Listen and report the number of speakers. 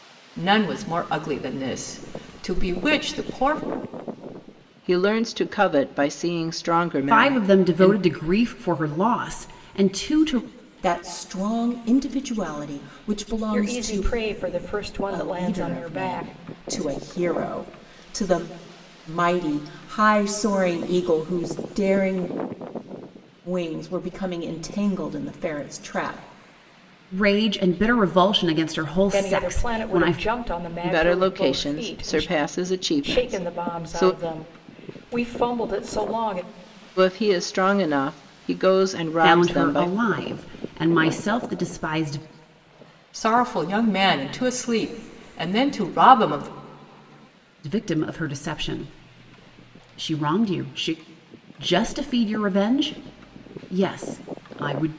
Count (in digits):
5